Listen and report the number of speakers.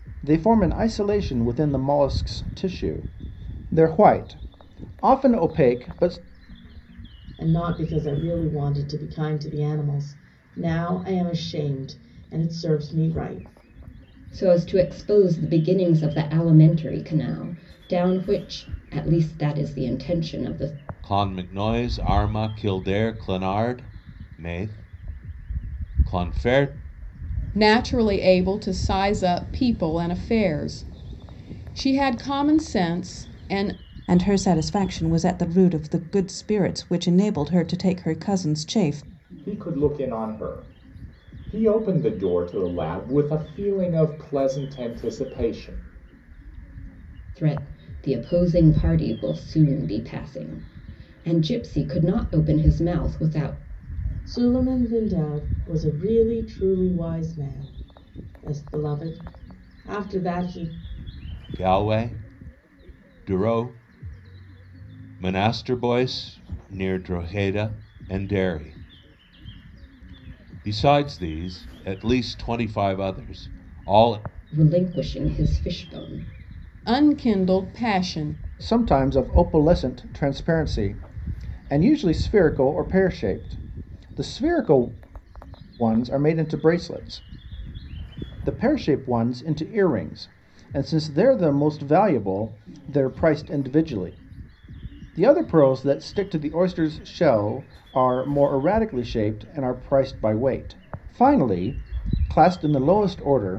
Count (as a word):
seven